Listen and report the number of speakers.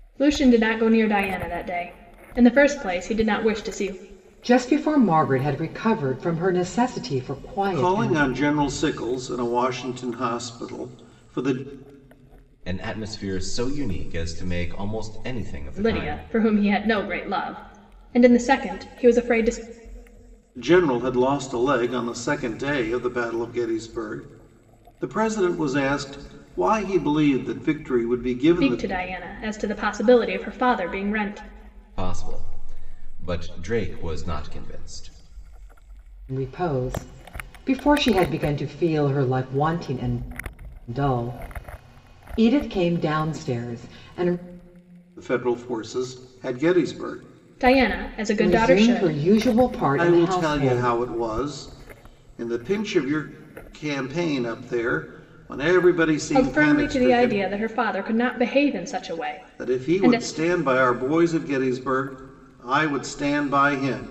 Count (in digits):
4